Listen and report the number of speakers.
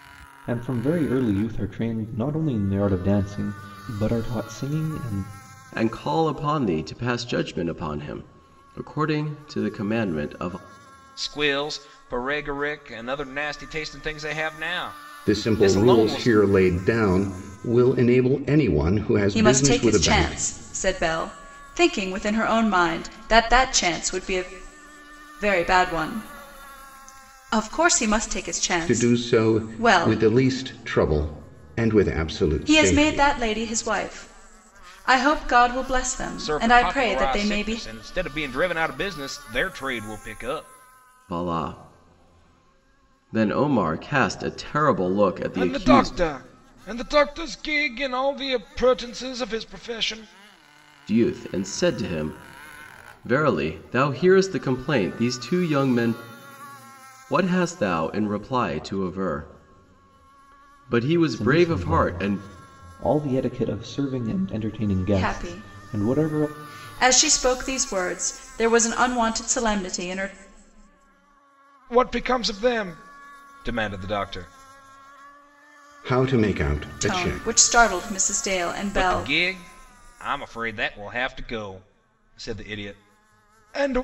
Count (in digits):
5